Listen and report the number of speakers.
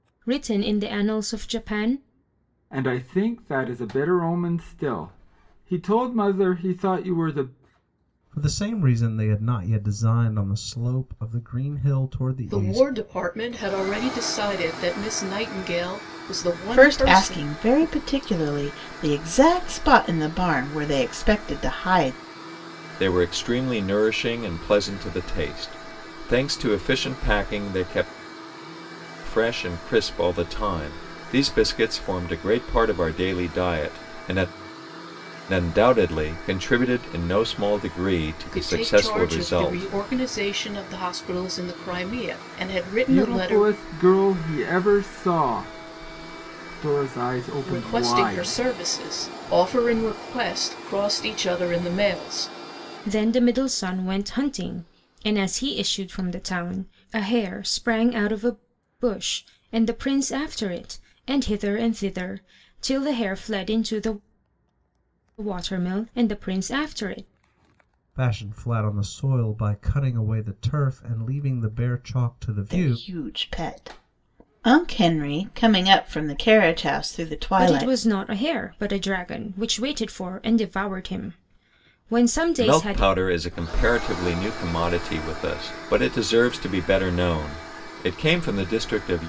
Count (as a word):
six